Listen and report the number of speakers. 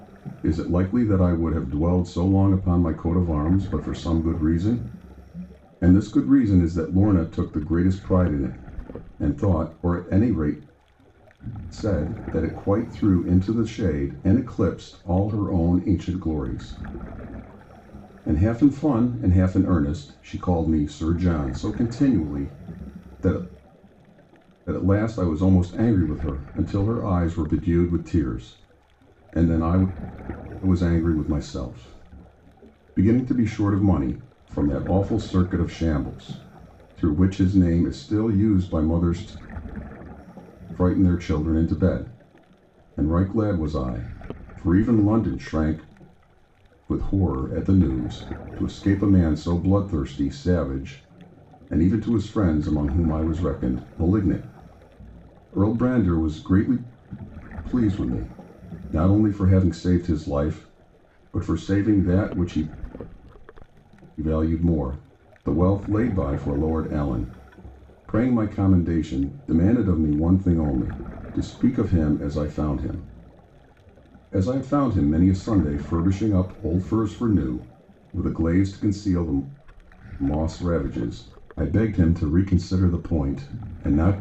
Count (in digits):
1